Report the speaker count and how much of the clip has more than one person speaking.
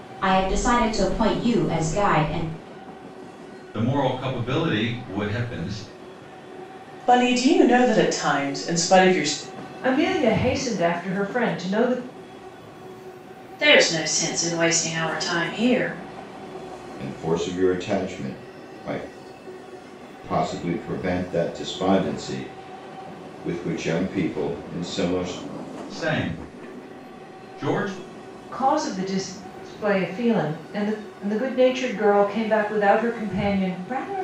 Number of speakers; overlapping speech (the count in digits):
6, no overlap